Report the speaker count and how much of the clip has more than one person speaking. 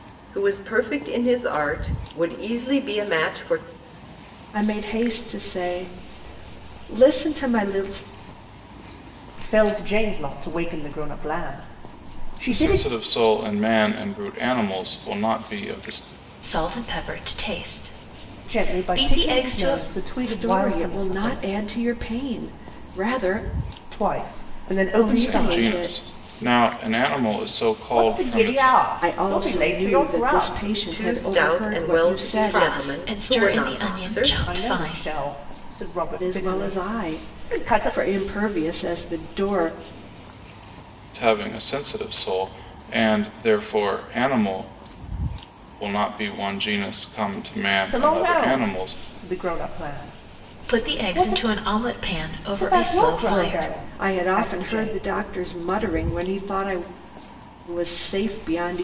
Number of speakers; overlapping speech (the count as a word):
five, about 29%